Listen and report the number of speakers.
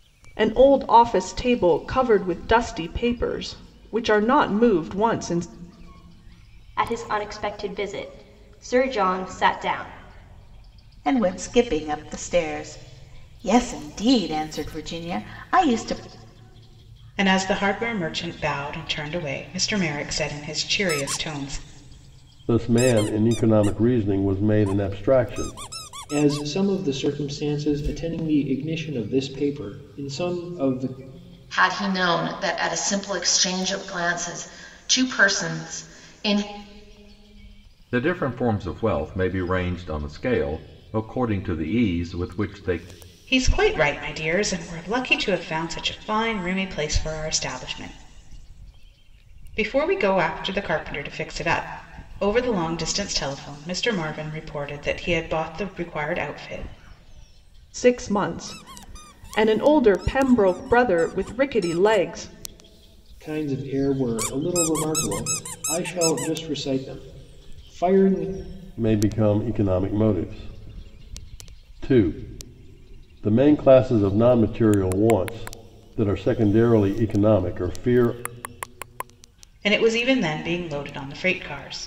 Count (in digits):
8